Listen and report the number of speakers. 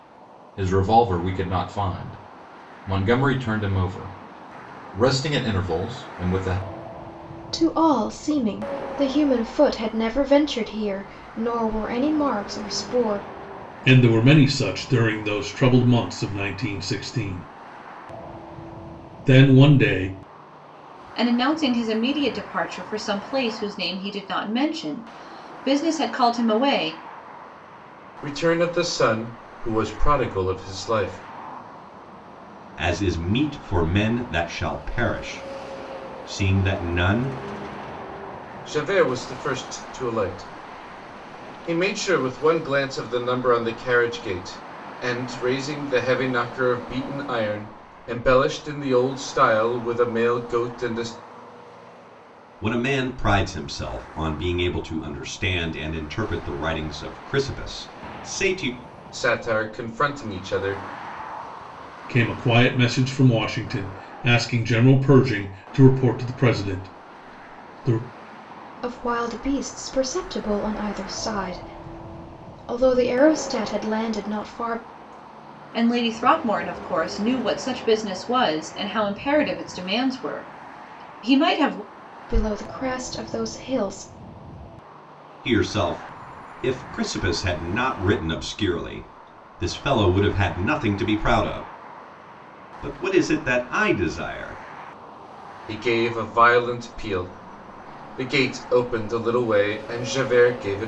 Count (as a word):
six